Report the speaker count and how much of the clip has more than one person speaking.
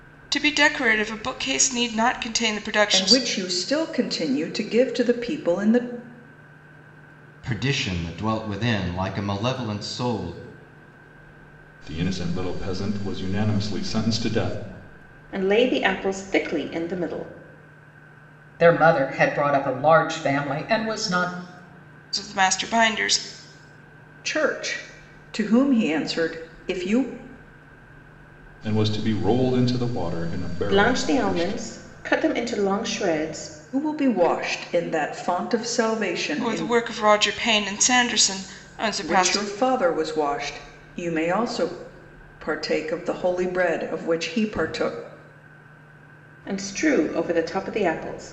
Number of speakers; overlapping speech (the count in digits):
6, about 4%